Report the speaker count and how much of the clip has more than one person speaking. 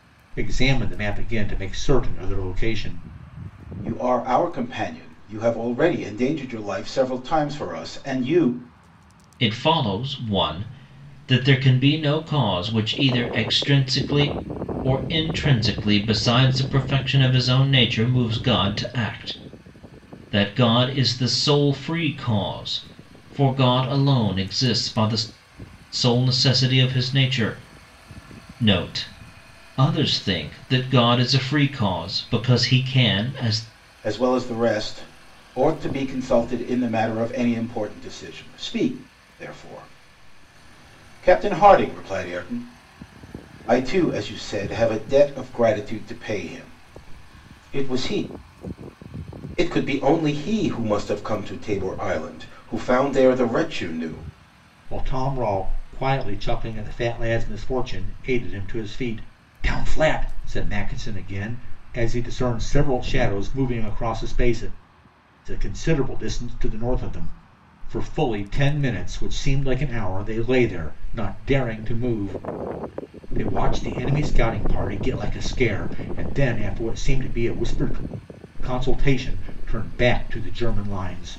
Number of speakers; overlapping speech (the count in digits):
3, no overlap